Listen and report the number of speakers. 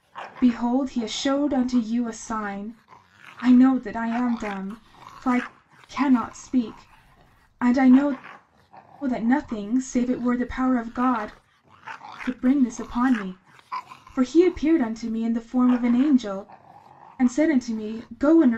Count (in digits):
1